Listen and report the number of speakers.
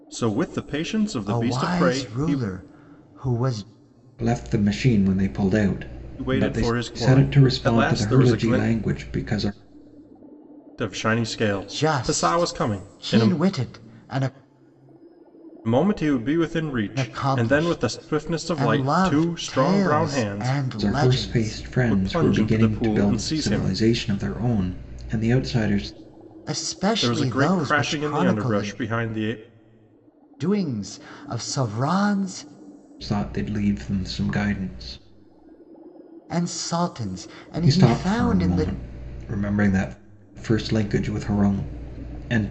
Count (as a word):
three